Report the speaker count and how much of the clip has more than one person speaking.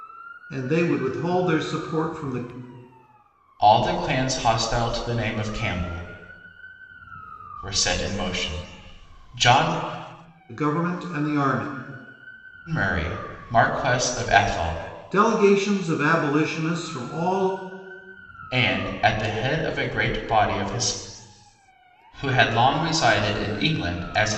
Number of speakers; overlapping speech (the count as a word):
two, no overlap